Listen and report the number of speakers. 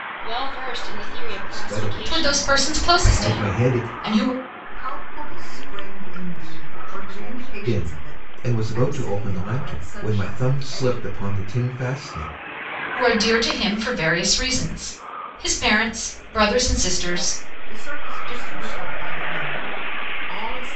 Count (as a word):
five